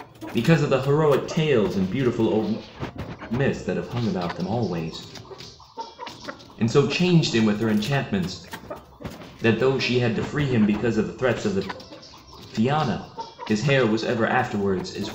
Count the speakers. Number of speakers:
one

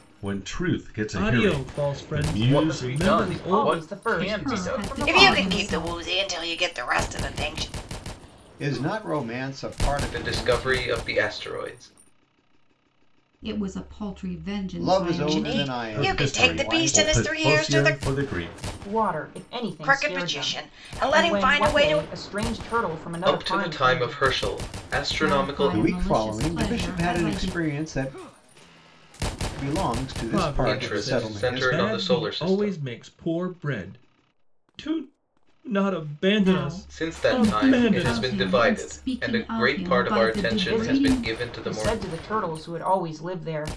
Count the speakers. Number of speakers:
eight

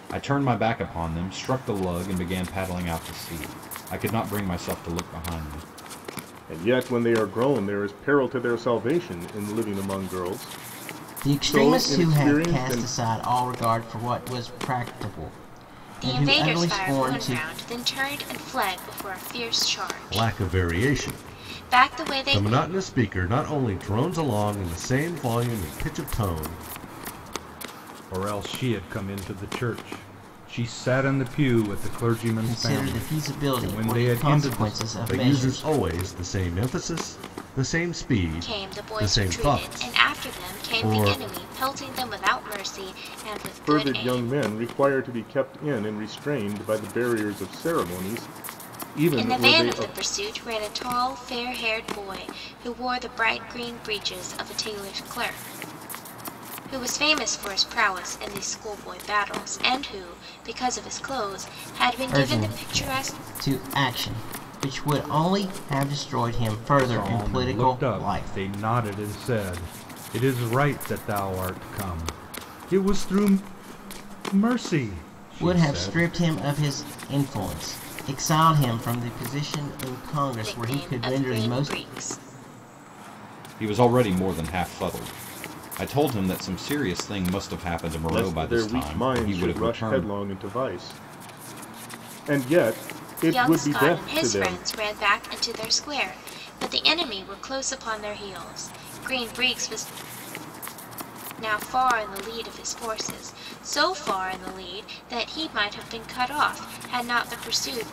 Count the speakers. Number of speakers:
six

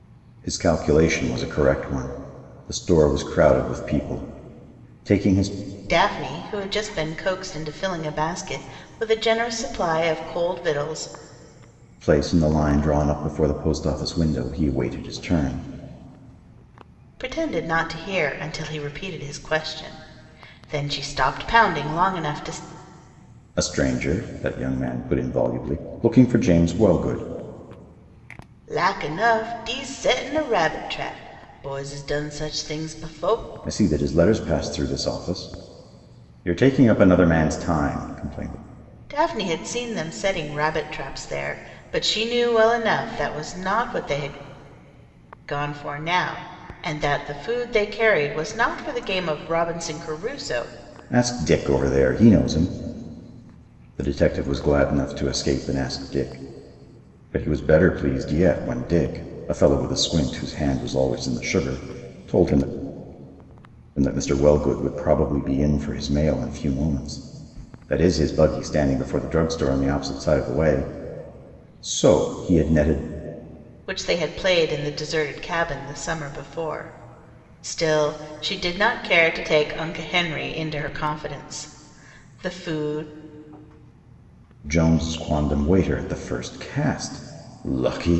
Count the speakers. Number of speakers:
two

